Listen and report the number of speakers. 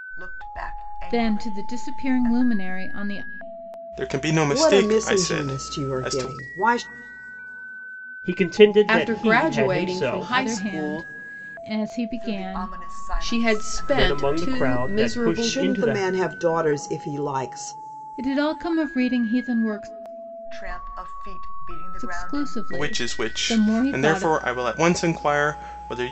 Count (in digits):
6